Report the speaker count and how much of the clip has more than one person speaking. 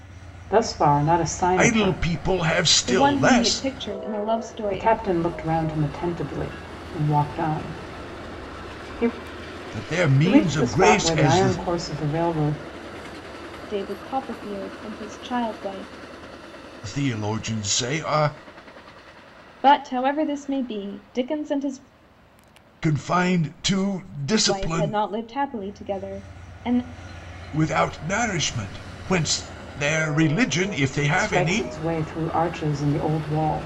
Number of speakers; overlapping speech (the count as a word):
three, about 12%